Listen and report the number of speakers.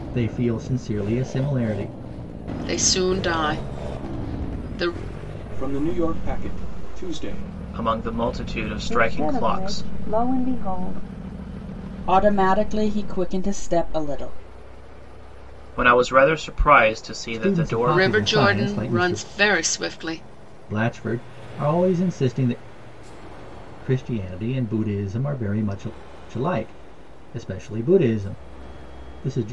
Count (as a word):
six